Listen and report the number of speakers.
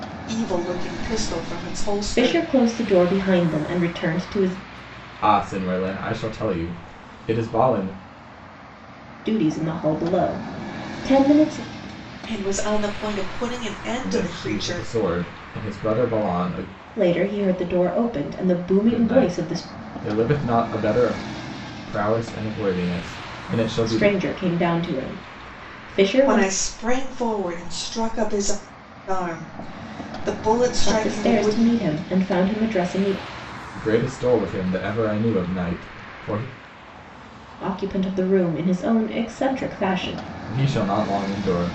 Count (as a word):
three